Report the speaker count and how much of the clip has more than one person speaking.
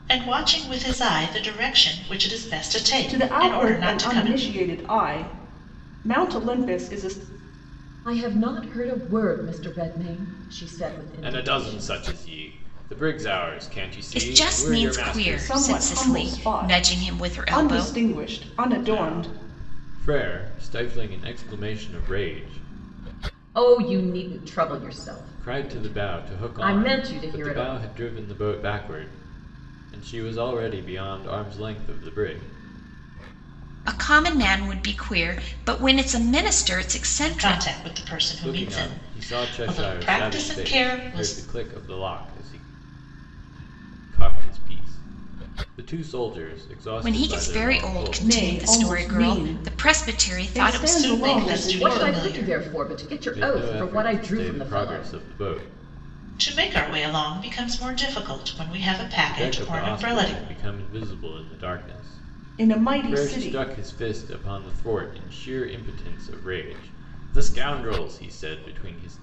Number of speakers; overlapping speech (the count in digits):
5, about 32%